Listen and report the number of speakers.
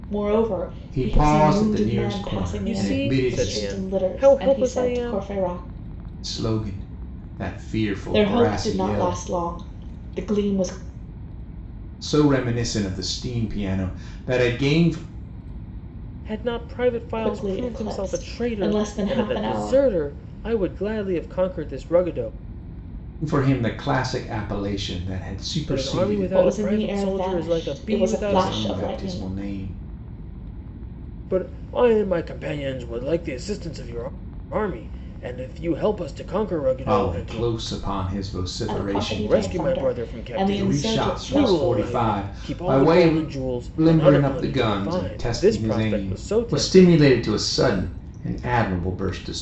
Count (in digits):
3